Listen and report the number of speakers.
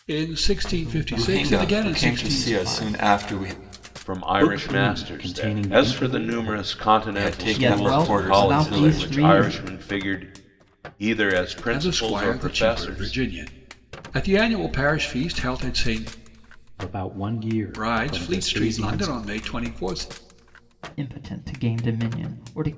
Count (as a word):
five